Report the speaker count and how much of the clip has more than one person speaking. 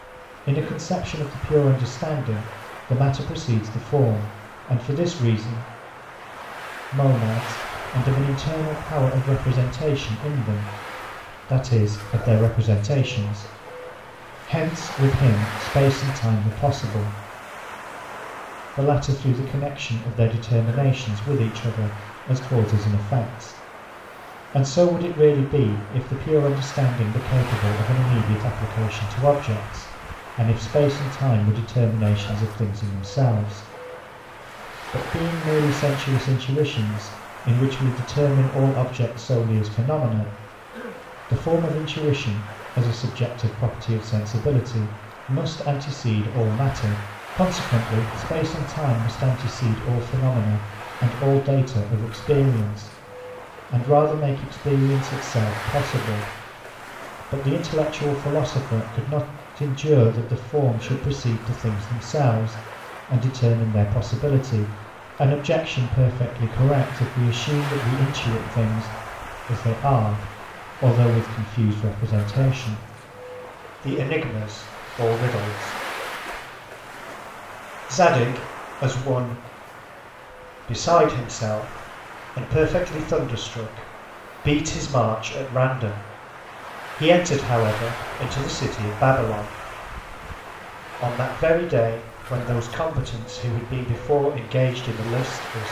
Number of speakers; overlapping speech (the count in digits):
1, no overlap